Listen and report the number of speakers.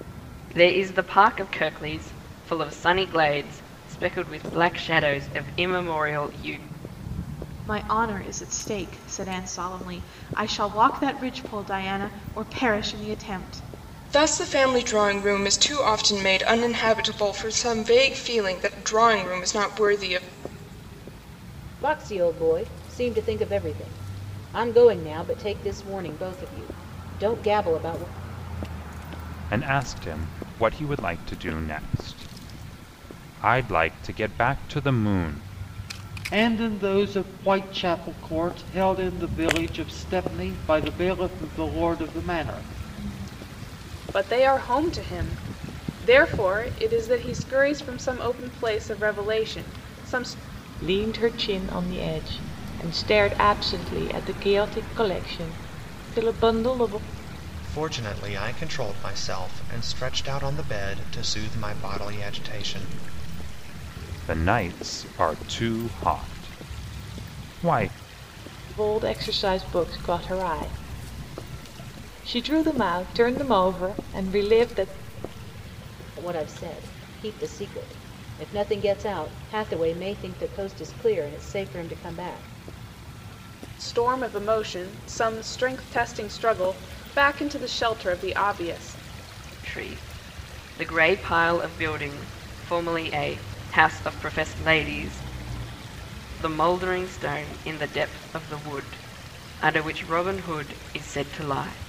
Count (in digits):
9